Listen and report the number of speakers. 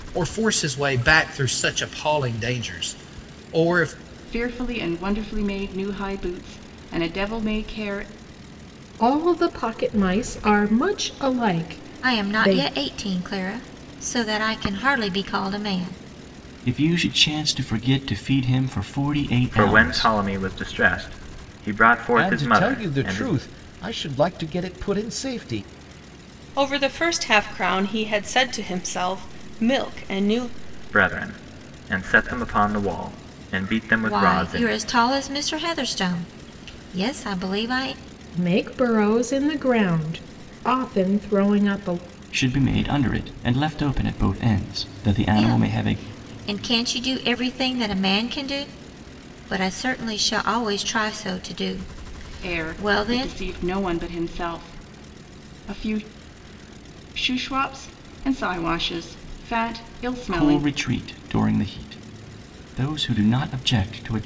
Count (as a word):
eight